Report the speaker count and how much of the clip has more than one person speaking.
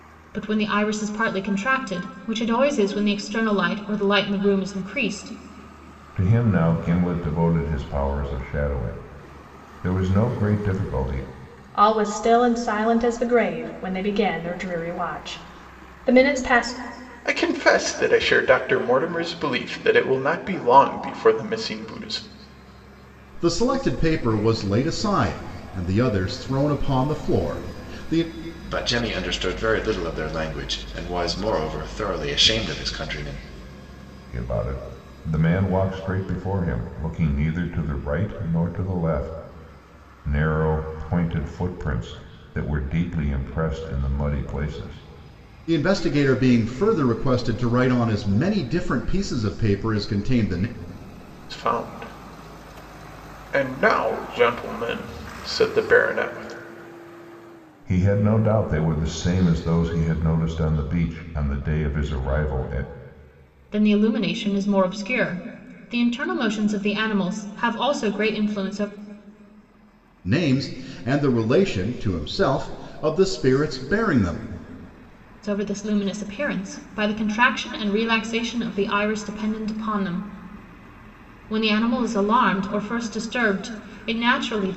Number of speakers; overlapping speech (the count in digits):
6, no overlap